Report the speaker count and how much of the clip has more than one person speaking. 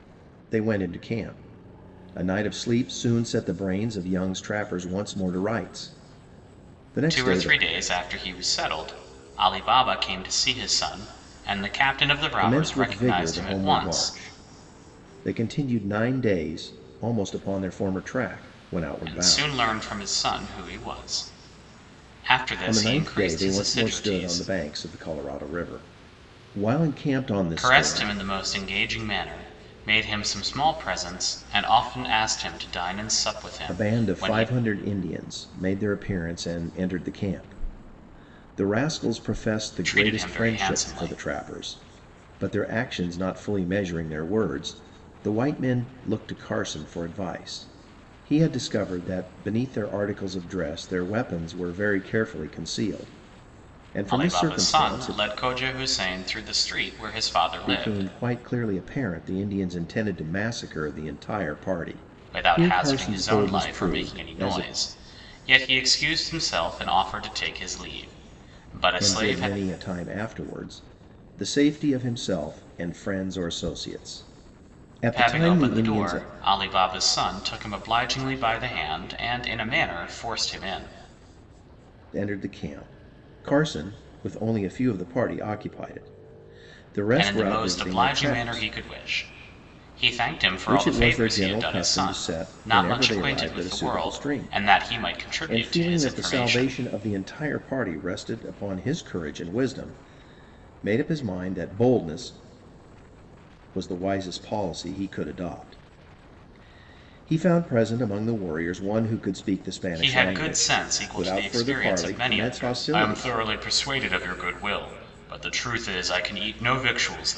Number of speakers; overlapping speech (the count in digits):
2, about 20%